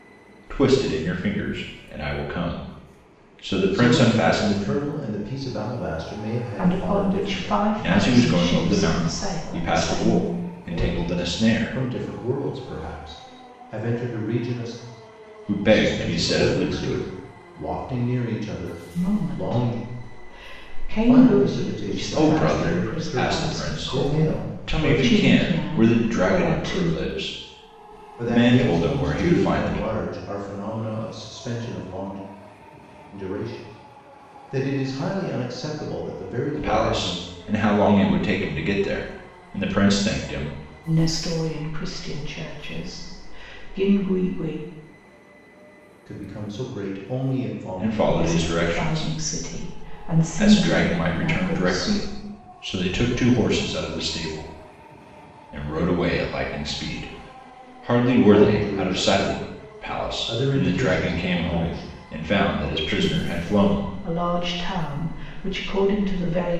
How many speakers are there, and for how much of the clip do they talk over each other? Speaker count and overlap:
three, about 36%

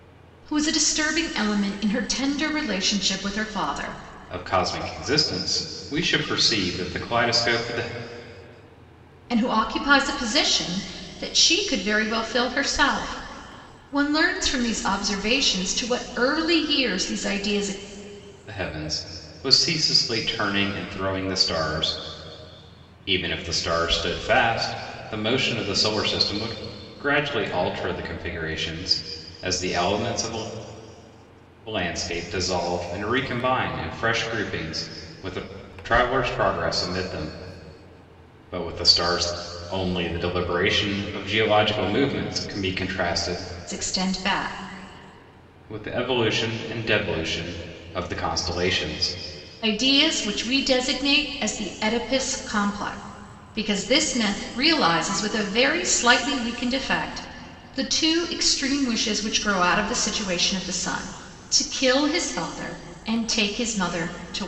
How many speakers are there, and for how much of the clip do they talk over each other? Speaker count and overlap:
two, no overlap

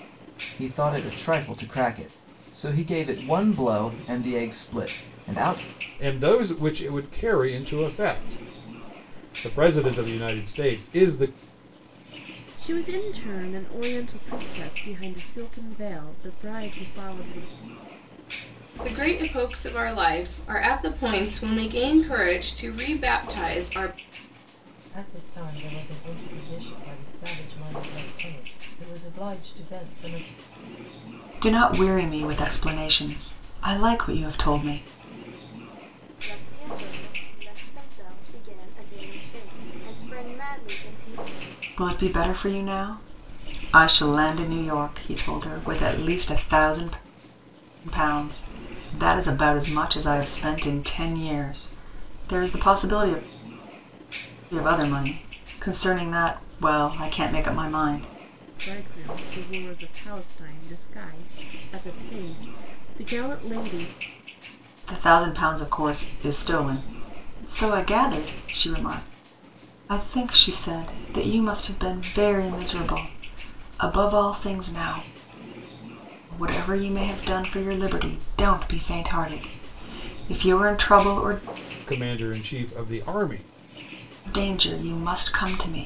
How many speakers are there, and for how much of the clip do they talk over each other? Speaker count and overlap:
seven, no overlap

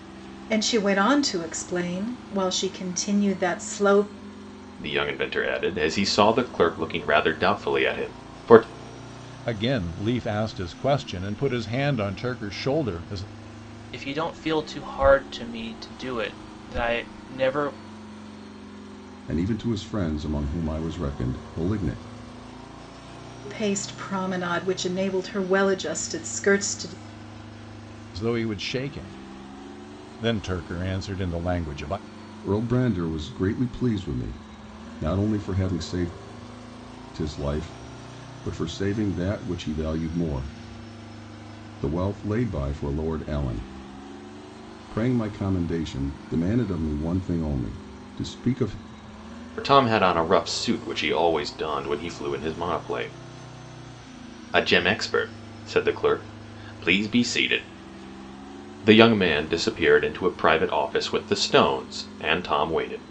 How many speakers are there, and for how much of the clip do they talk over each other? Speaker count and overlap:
five, no overlap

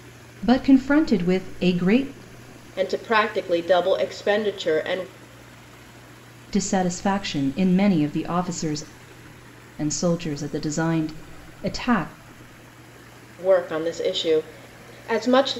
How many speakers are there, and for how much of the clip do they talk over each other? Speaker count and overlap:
two, no overlap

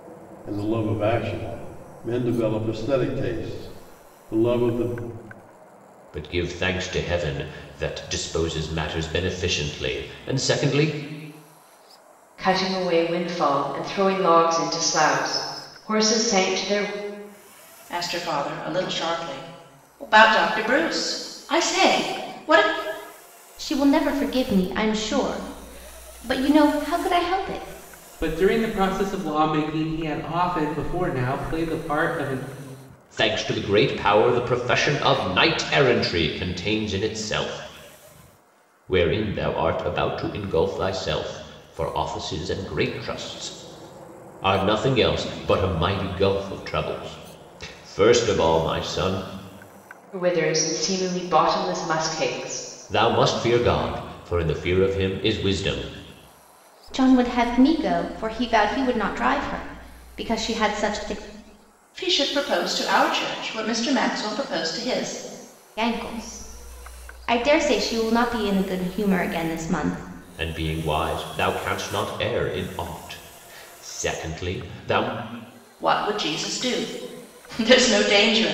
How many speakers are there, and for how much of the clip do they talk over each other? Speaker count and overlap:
six, no overlap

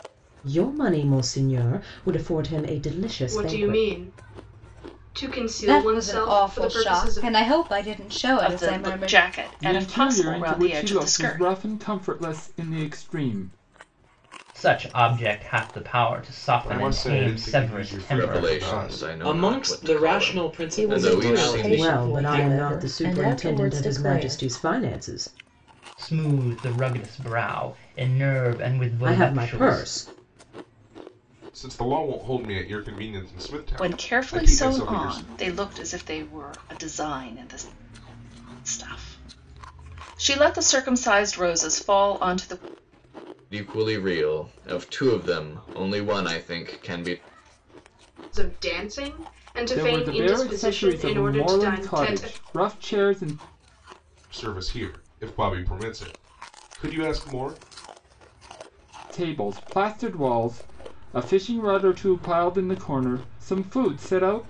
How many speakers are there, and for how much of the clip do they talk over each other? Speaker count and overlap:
ten, about 28%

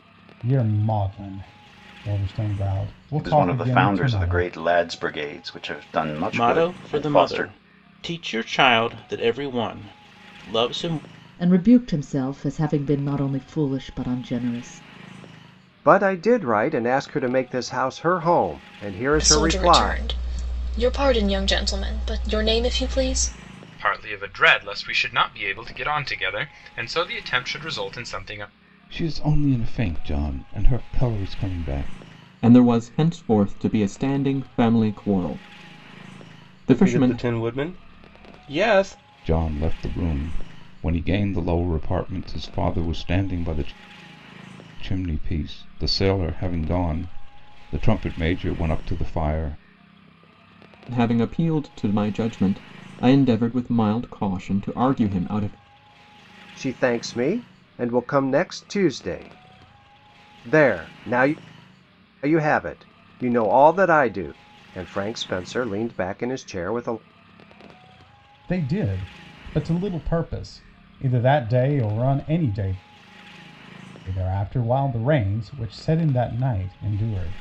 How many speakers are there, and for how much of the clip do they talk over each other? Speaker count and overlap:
ten, about 5%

